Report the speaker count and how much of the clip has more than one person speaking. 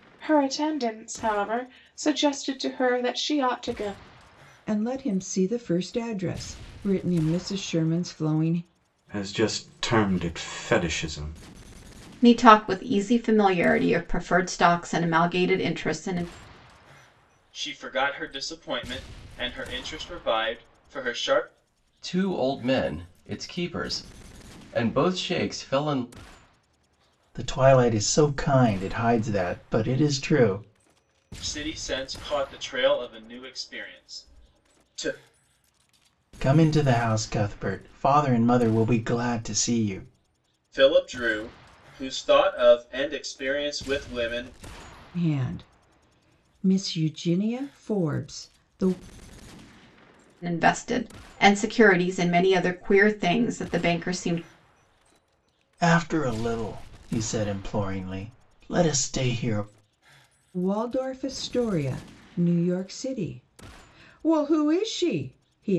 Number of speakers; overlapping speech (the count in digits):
7, no overlap